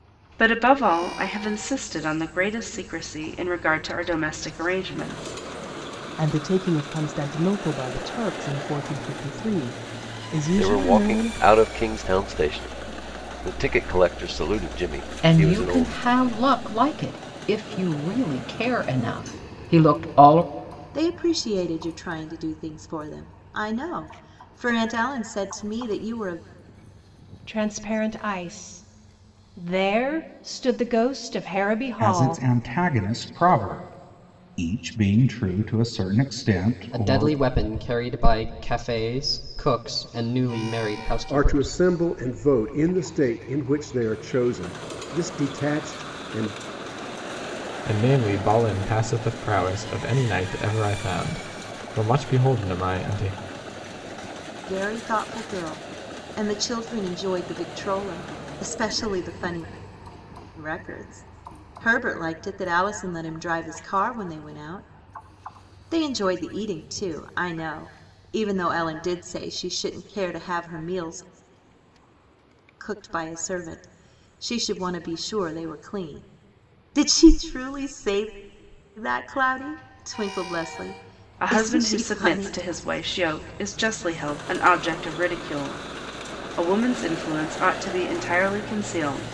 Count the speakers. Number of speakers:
ten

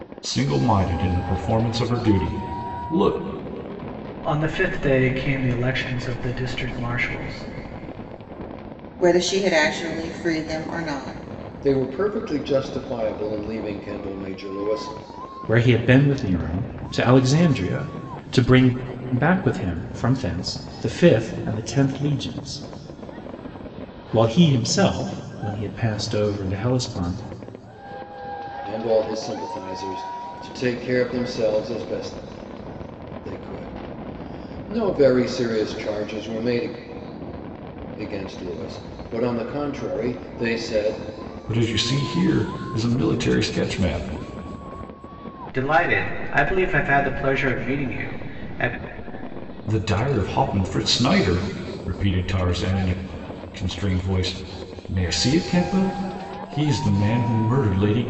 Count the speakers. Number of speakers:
five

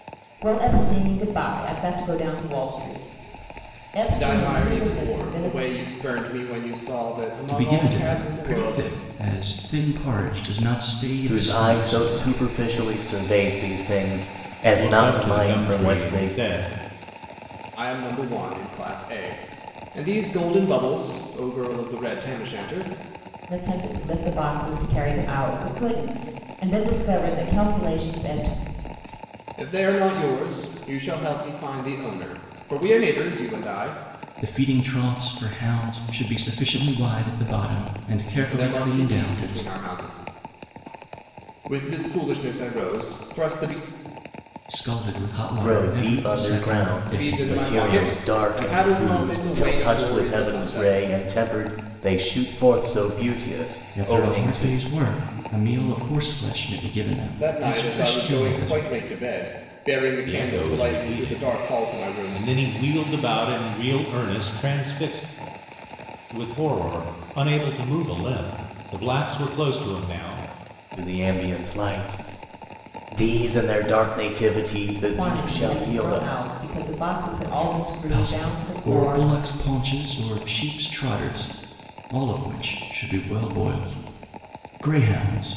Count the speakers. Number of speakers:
five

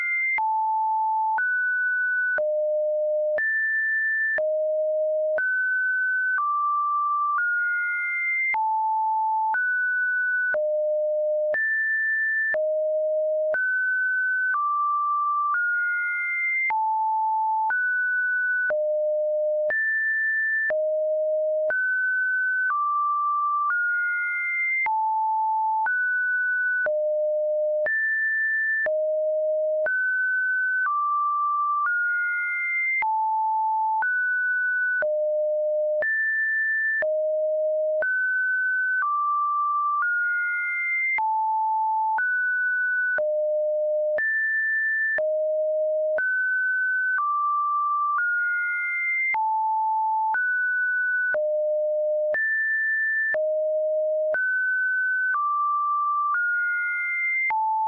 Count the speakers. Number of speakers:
zero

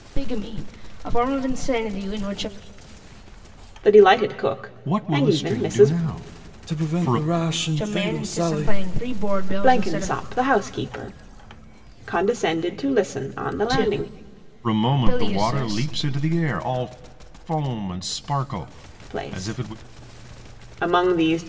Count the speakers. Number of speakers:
four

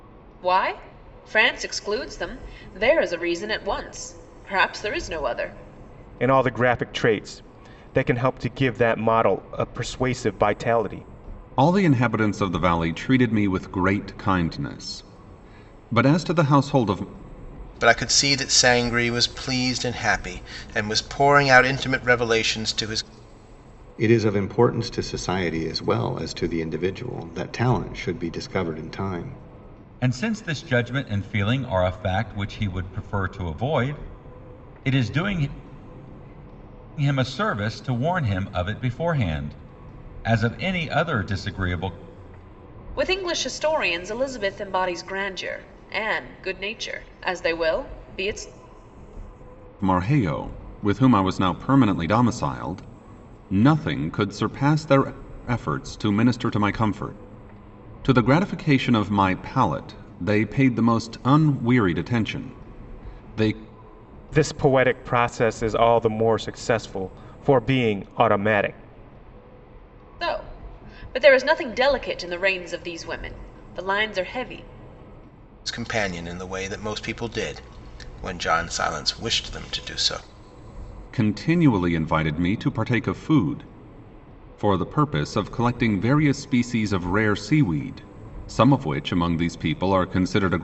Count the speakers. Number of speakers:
six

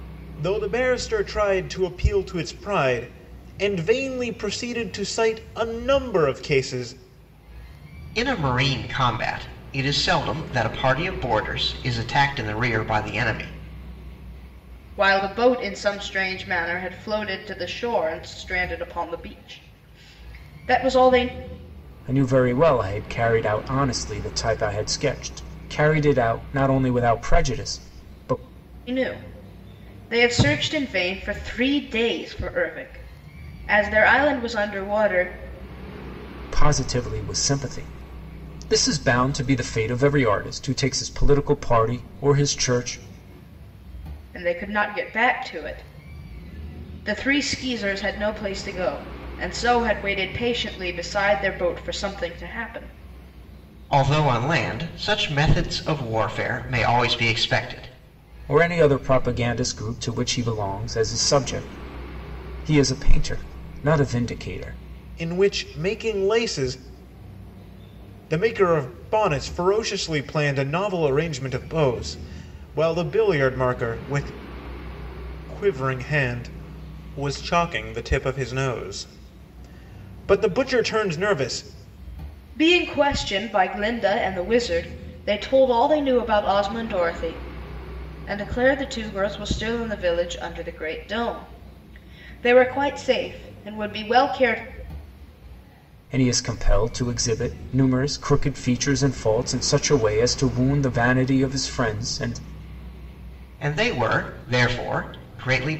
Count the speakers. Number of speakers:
four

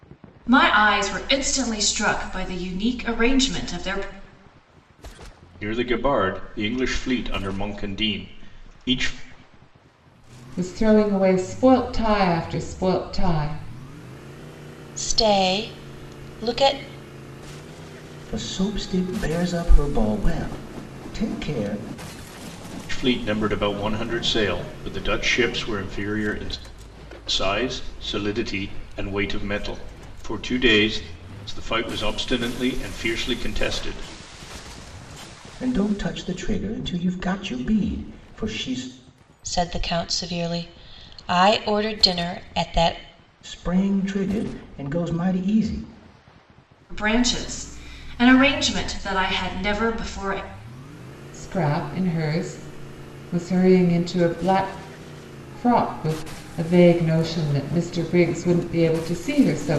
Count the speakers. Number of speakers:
five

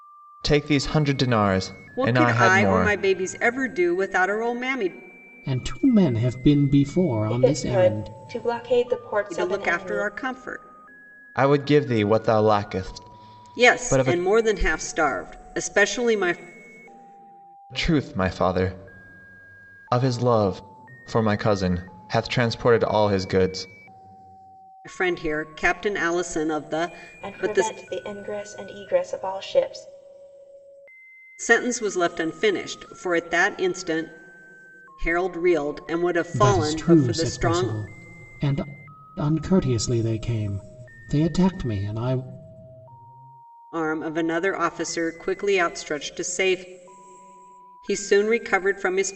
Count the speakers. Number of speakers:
four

